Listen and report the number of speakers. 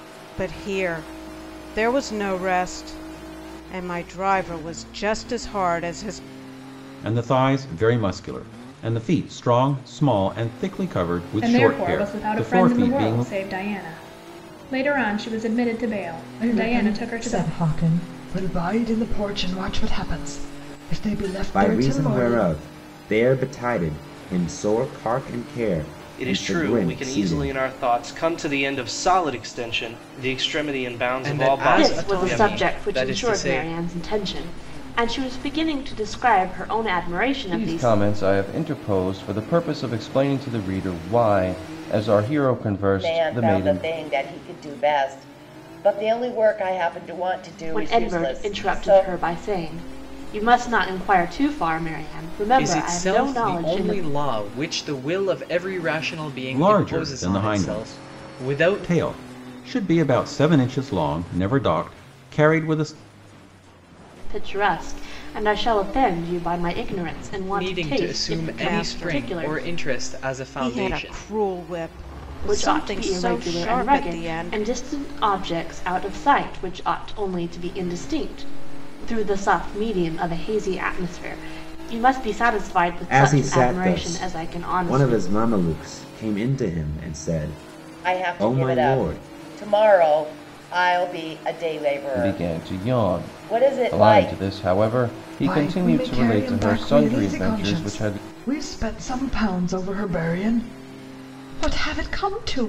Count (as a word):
ten